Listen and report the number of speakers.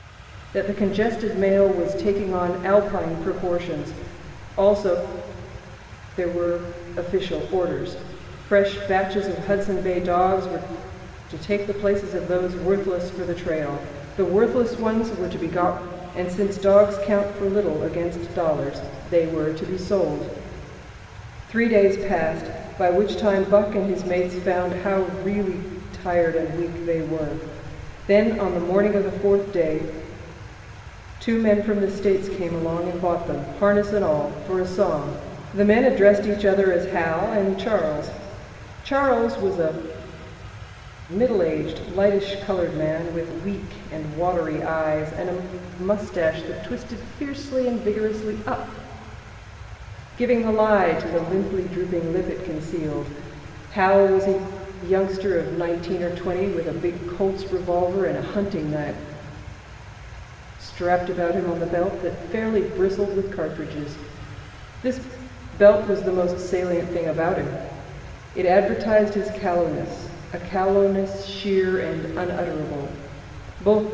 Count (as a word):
one